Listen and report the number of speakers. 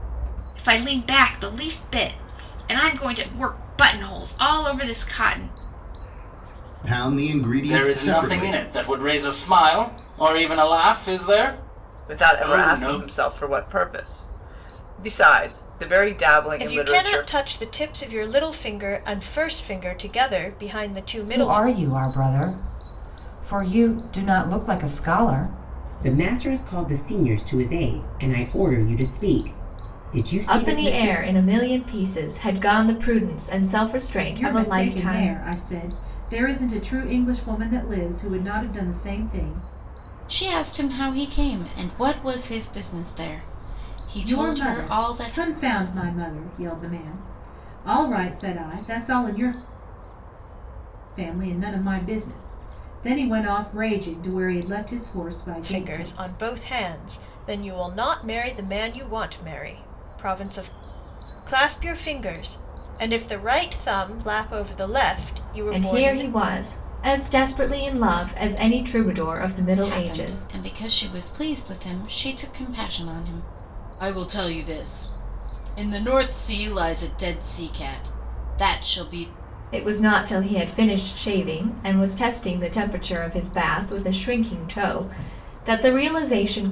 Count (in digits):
10